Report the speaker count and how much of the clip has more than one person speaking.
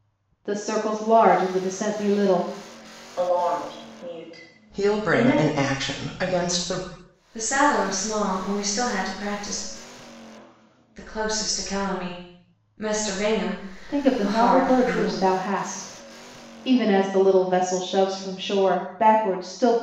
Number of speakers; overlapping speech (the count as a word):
four, about 11%